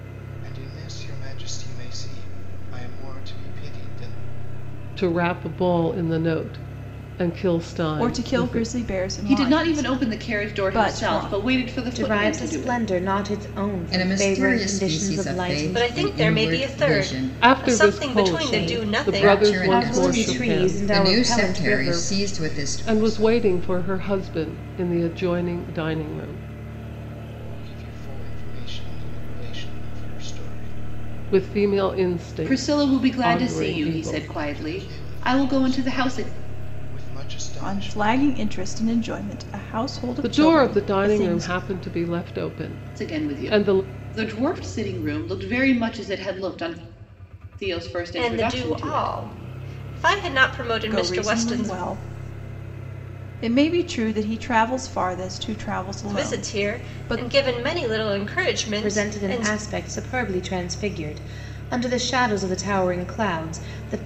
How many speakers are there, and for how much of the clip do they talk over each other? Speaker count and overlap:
7, about 38%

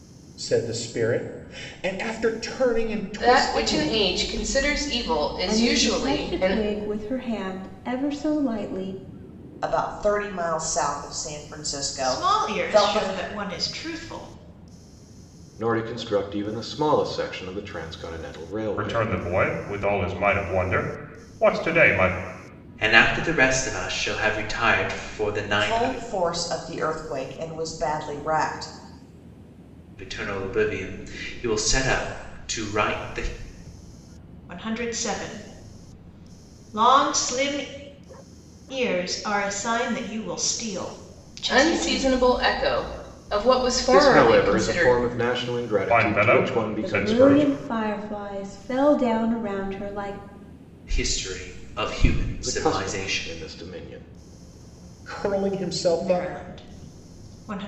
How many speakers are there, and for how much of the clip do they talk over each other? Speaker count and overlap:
8, about 15%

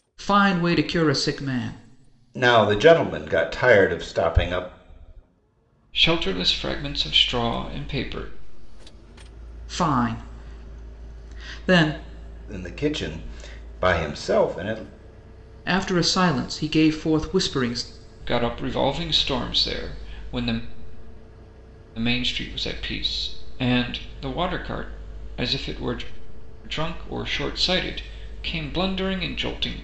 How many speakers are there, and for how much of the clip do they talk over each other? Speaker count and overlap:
3, no overlap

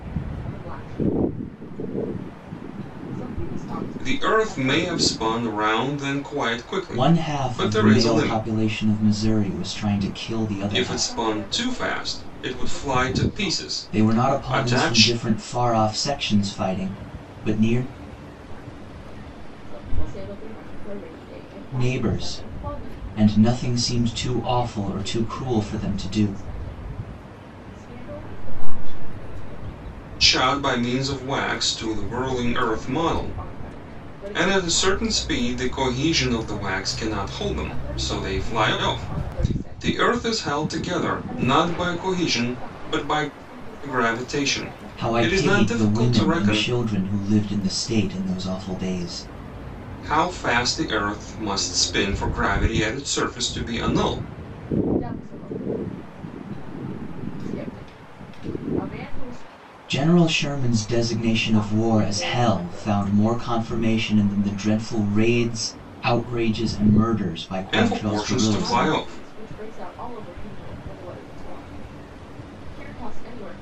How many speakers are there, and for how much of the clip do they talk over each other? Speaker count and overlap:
3, about 40%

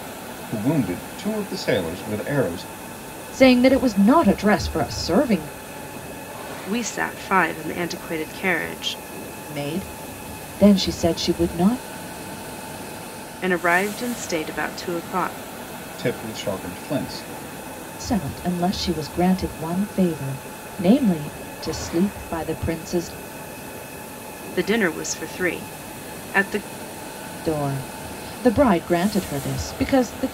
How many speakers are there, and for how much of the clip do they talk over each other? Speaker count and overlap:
3, no overlap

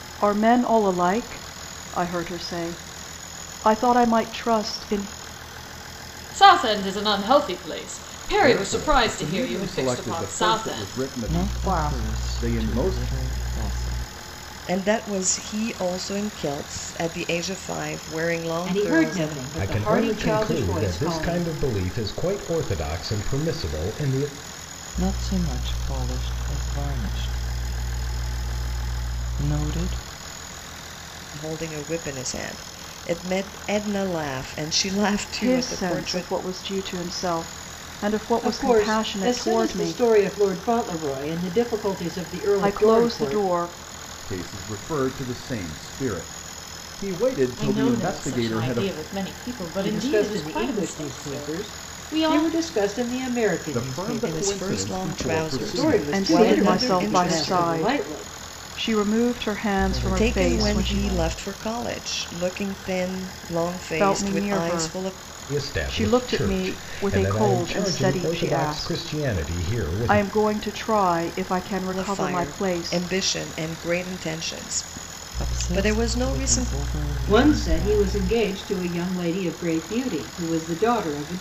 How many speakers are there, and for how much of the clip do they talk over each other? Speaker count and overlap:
7, about 38%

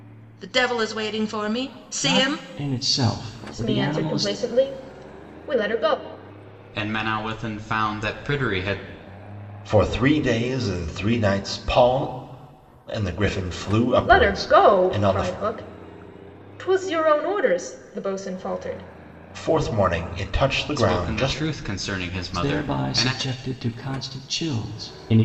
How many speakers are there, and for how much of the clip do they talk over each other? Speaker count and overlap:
5, about 16%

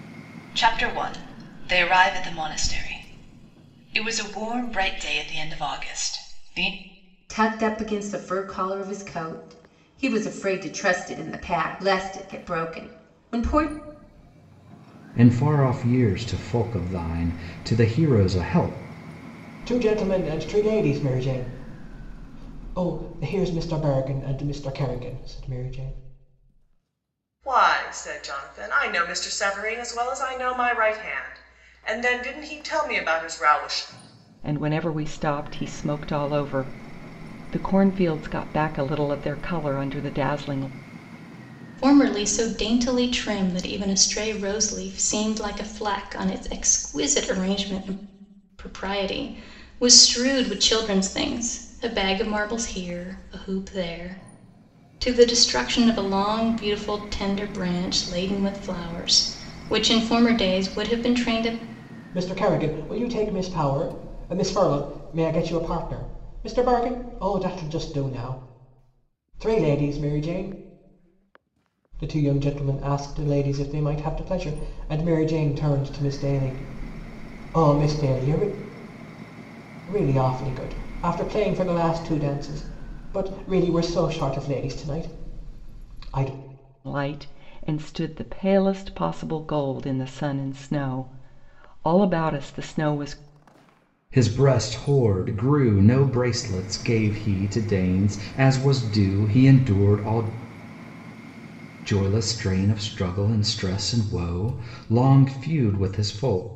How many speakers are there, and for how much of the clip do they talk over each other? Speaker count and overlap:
7, no overlap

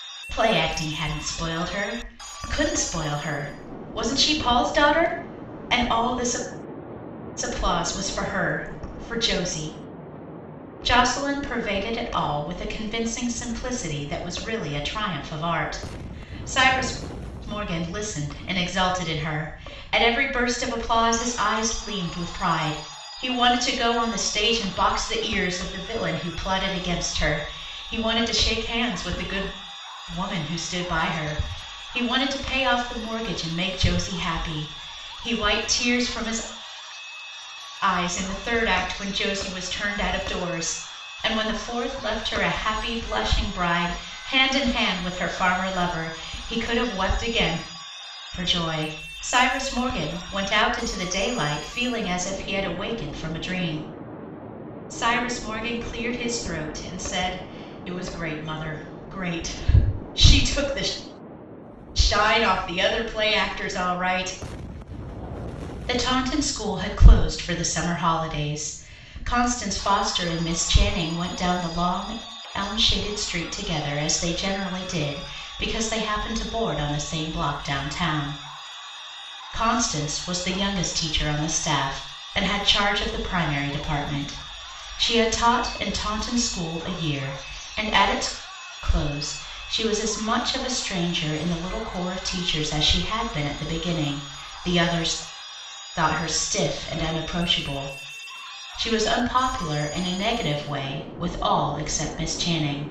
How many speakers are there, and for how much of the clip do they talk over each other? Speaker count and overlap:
1, no overlap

